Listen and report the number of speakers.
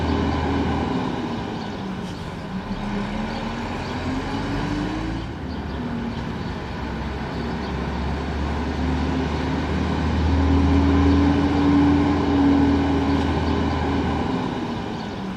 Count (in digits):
0